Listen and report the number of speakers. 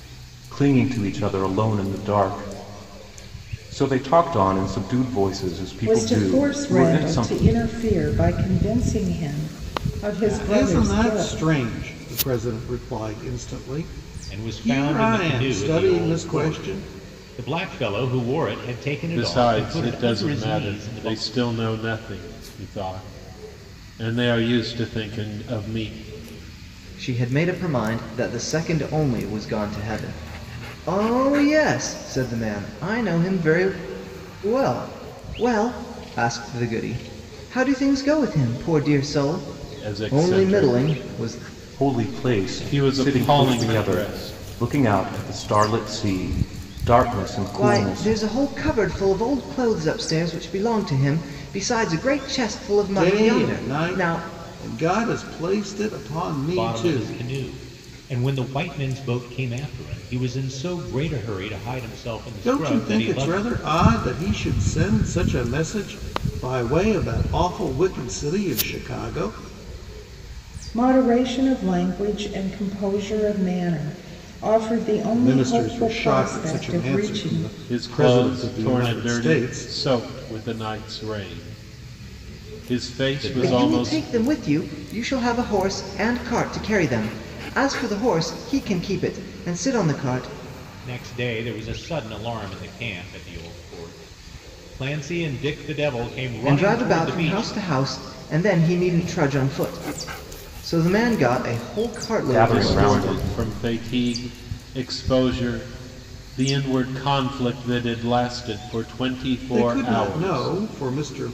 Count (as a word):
six